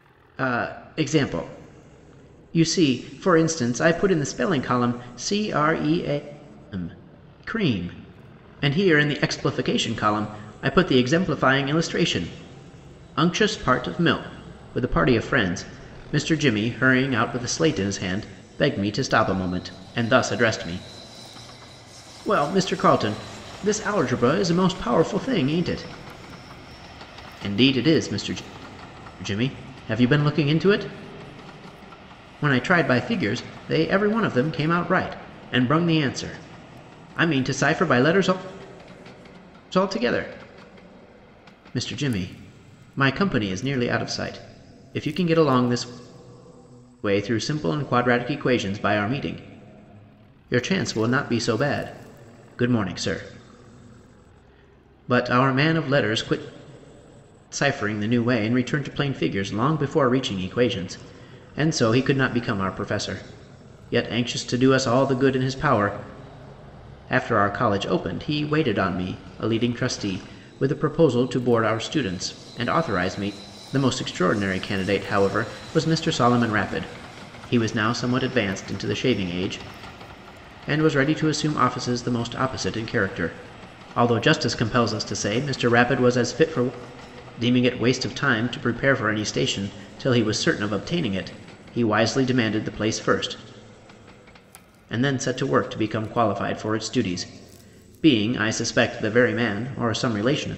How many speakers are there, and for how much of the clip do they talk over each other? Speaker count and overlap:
one, no overlap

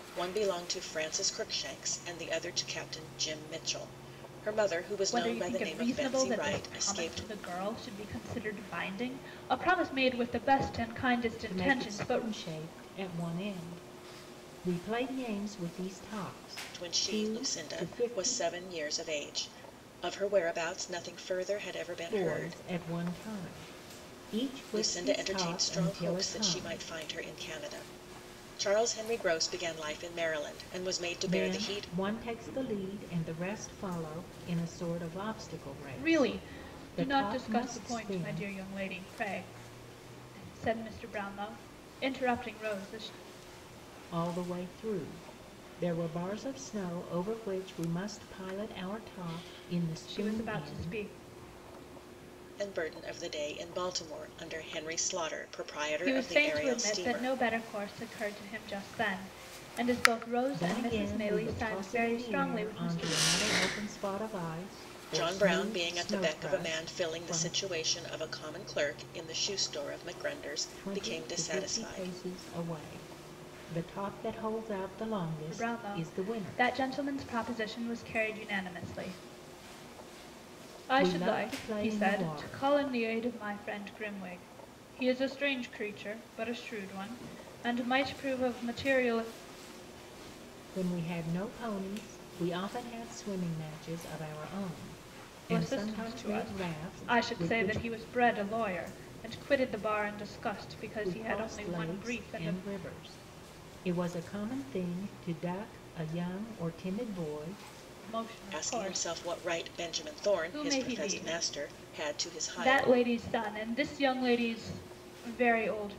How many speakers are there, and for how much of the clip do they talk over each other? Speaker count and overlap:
three, about 26%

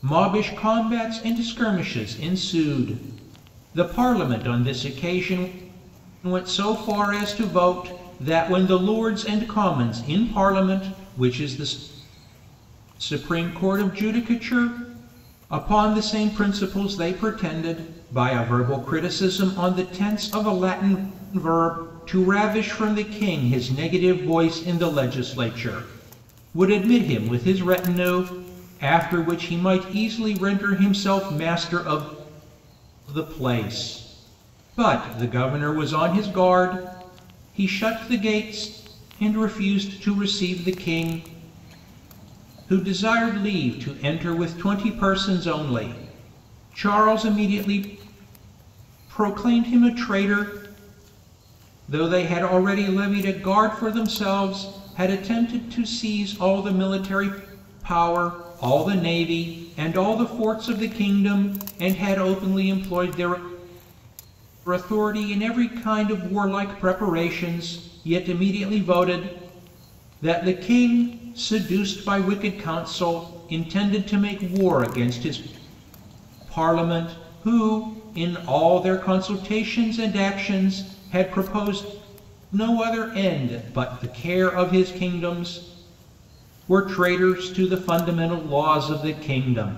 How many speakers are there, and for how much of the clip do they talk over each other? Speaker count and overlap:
one, no overlap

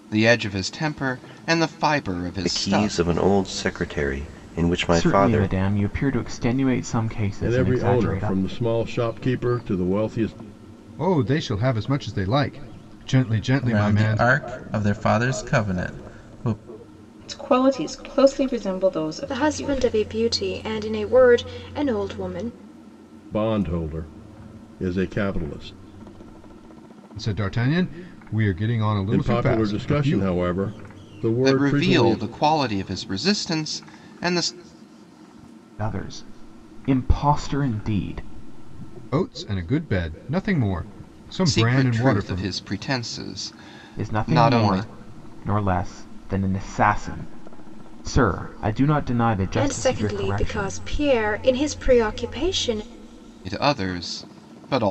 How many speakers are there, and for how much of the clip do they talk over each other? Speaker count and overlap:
eight, about 16%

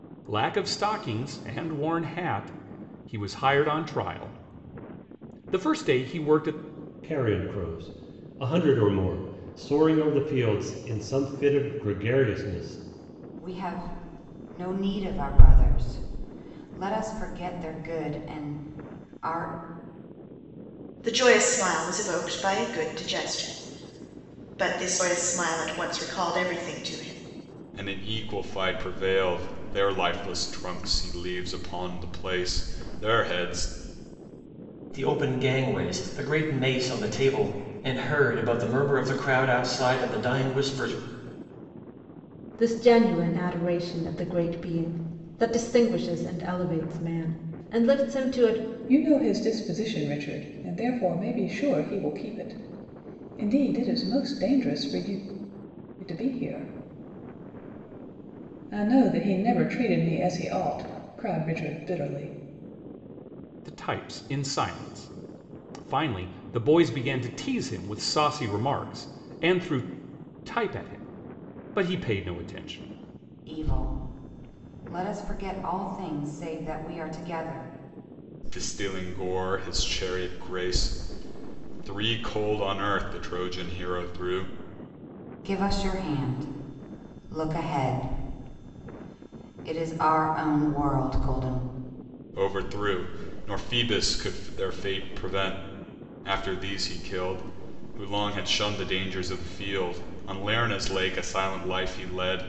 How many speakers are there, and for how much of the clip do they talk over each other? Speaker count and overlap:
eight, no overlap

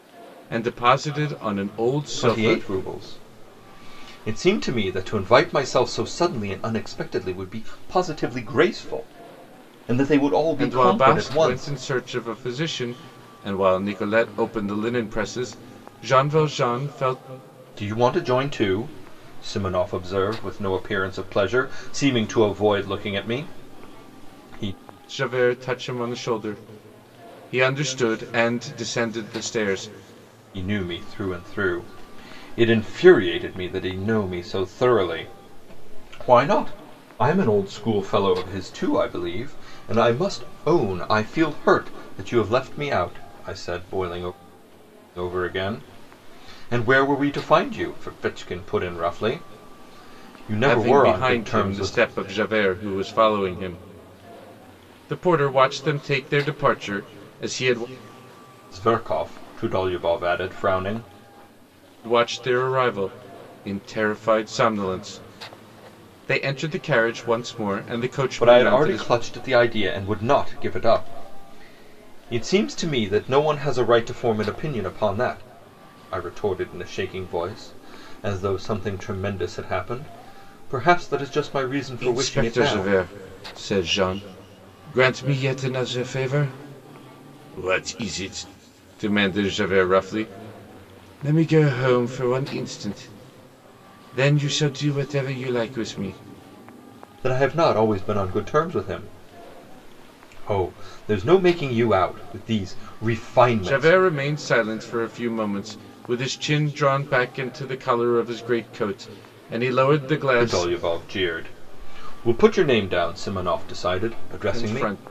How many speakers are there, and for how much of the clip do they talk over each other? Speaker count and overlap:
two, about 5%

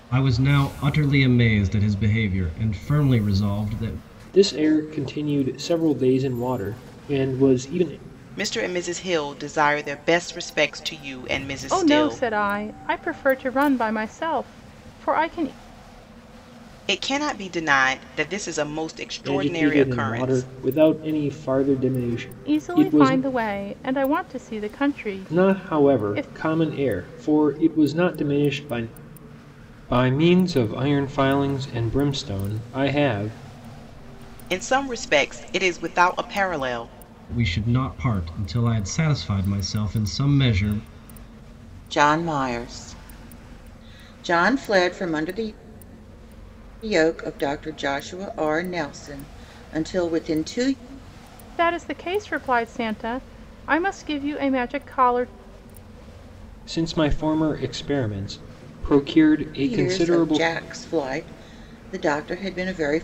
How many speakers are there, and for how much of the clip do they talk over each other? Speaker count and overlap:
four, about 7%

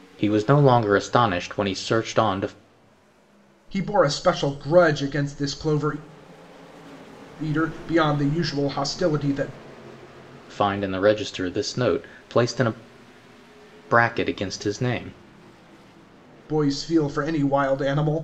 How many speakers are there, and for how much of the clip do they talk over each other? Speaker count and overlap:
two, no overlap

